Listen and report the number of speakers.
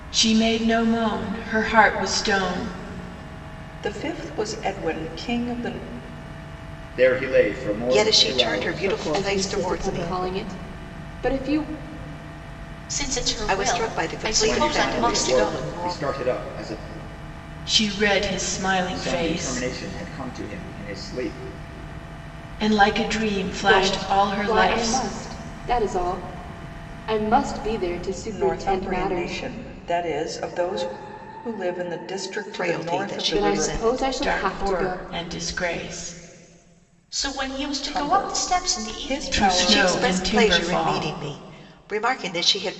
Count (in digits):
7